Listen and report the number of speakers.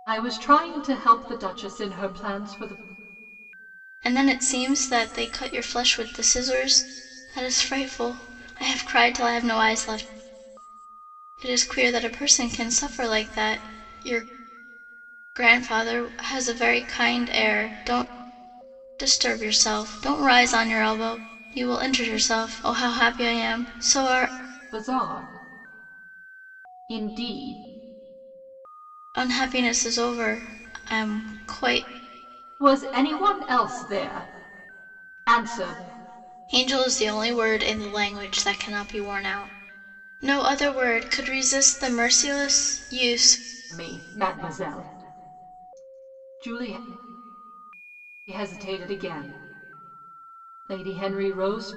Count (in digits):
2